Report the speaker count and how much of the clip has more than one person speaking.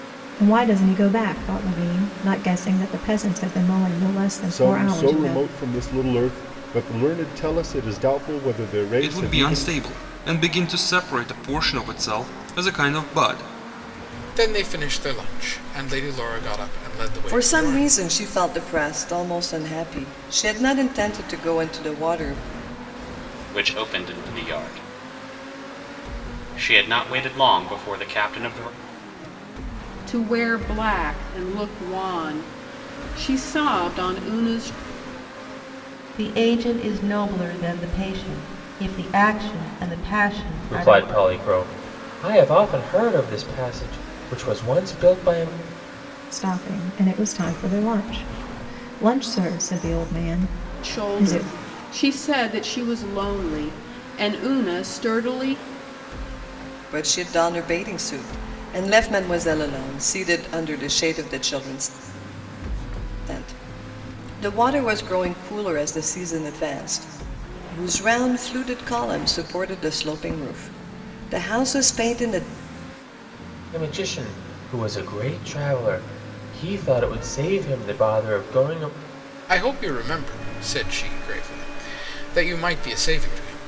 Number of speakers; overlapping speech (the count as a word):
nine, about 4%